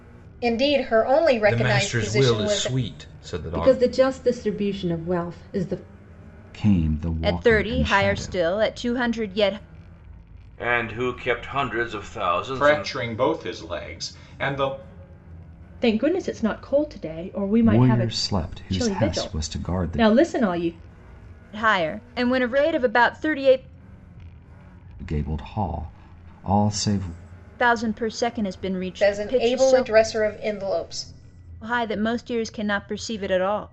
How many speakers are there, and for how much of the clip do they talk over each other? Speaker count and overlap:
eight, about 18%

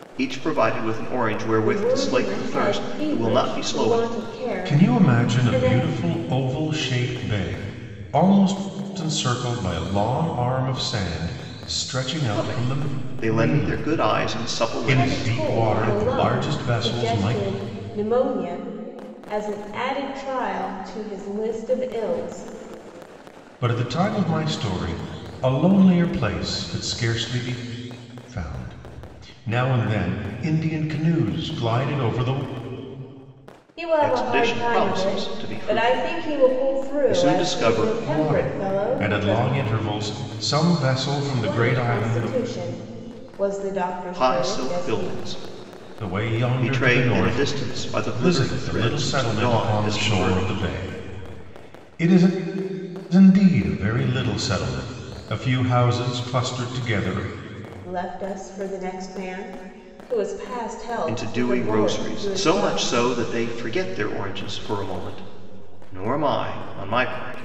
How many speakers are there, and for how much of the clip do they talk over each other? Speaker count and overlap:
three, about 31%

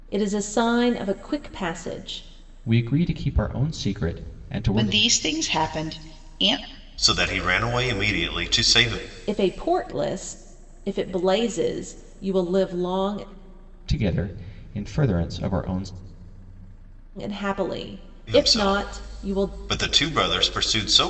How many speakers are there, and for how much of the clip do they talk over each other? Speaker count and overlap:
four, about 8%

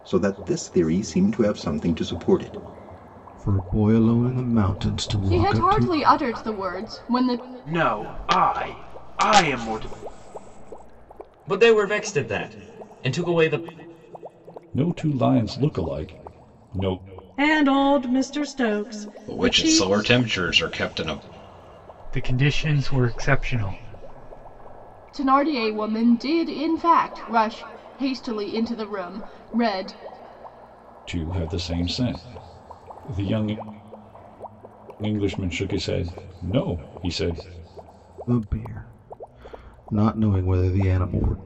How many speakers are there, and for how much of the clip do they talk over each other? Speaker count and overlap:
nine, about 3%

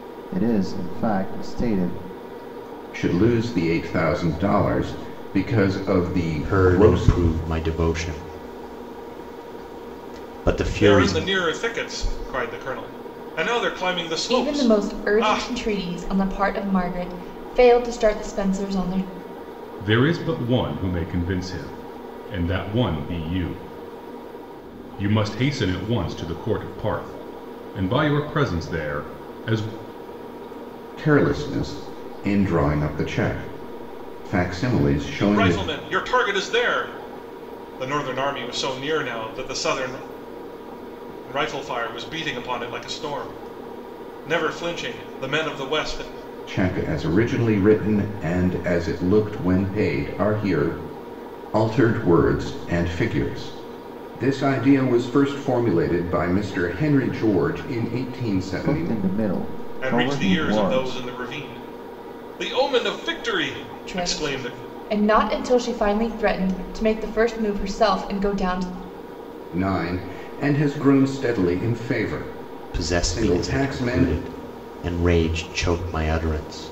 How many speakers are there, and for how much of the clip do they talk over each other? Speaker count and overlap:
six, about 9%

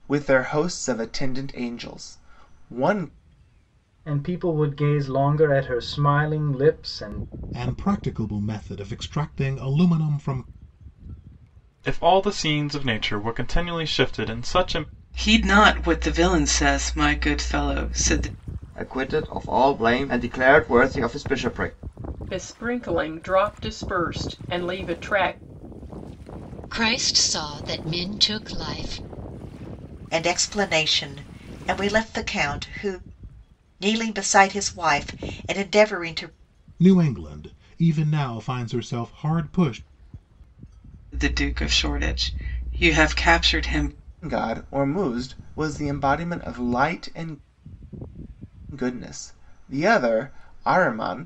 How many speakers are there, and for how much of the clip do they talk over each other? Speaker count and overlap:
nine, no overlap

